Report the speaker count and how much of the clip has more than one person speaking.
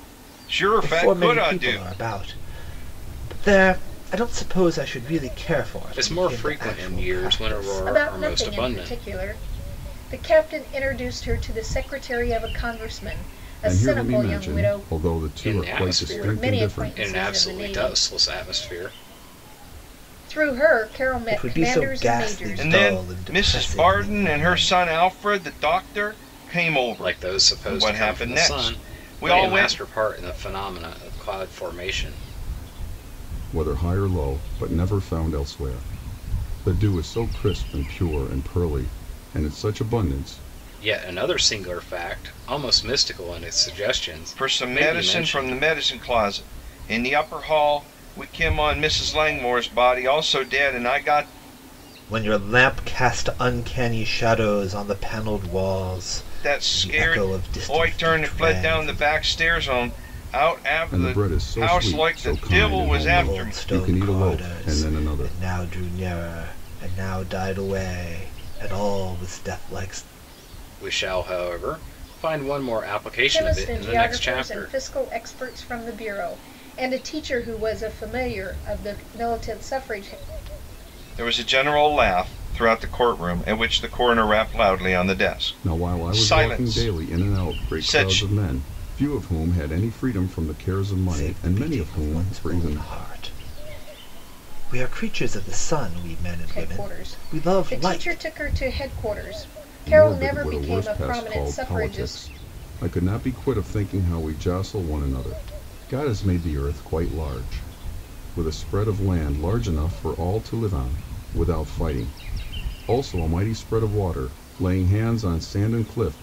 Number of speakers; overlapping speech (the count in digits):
5, about 29%